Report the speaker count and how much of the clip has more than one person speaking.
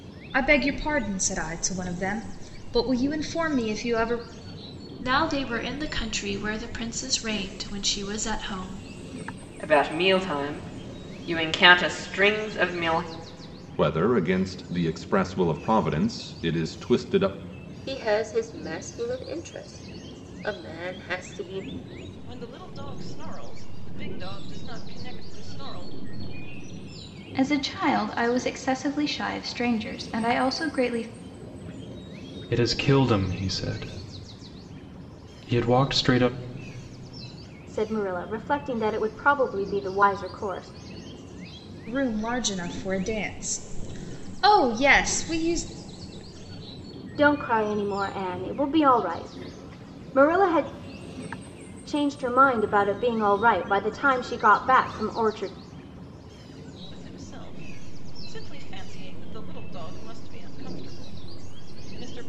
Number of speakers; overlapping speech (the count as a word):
nine, no overlap